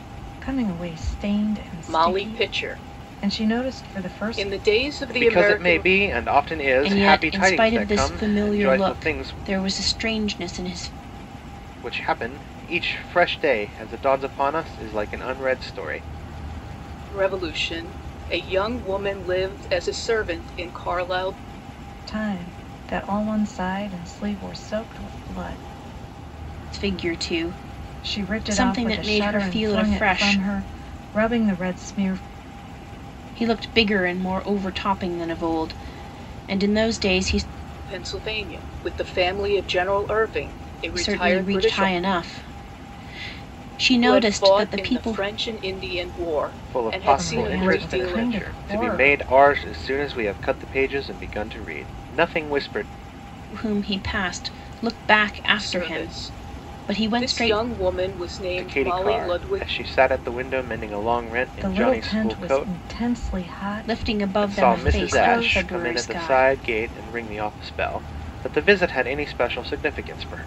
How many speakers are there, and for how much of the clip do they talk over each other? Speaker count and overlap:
4, about 29%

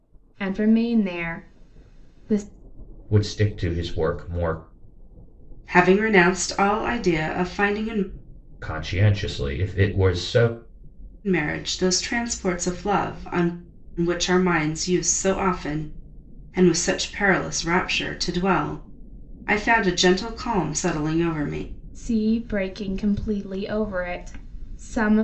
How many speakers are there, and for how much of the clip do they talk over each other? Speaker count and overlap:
3, no overlap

